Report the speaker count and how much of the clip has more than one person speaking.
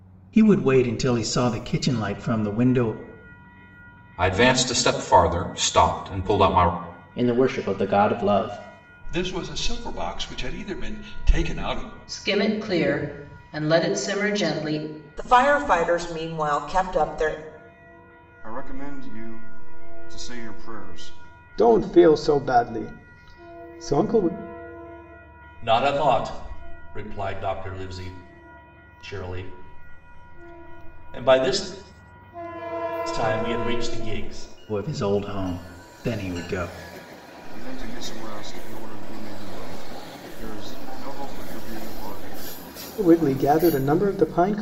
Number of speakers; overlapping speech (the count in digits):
9, no overlap